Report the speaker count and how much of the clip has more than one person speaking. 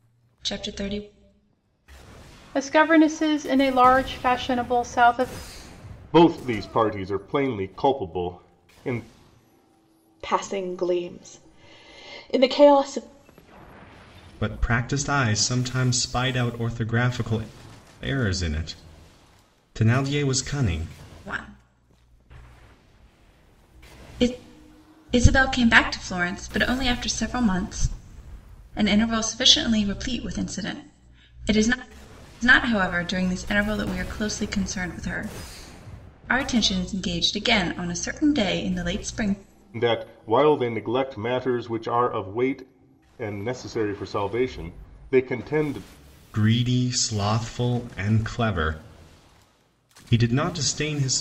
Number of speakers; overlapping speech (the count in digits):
5, no overlap